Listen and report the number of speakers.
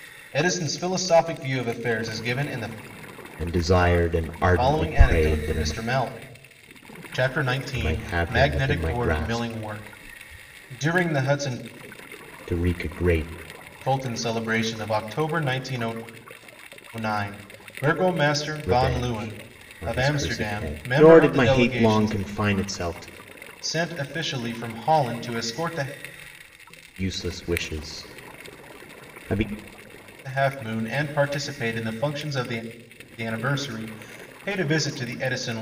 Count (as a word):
two